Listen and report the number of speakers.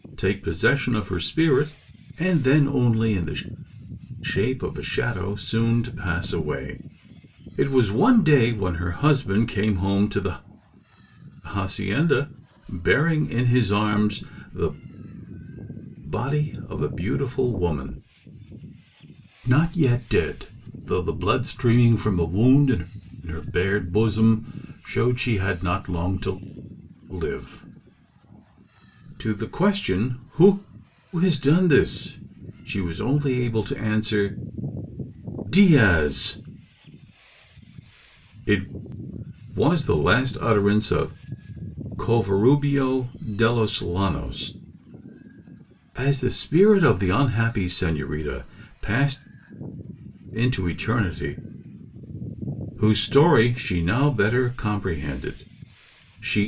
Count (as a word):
one